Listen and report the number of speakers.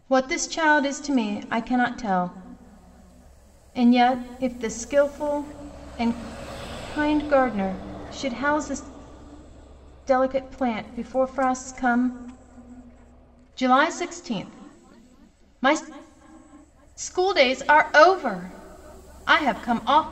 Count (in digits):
1